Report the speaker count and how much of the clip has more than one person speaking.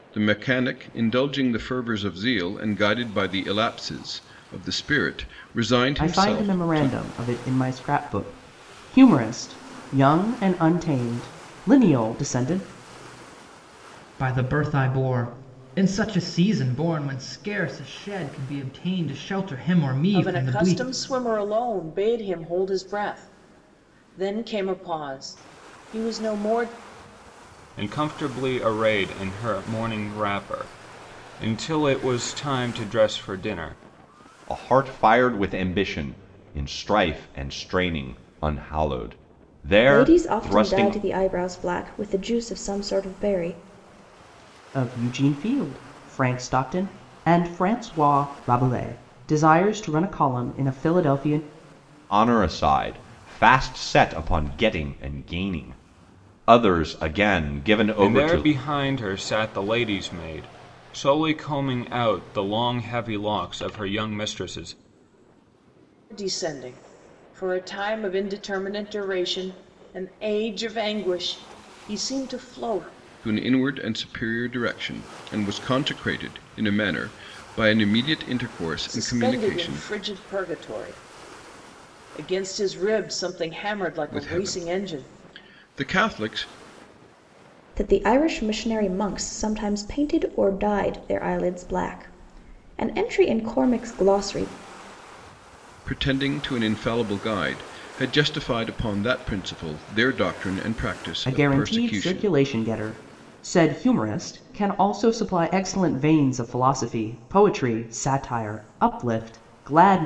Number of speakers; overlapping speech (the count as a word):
seven, about 6%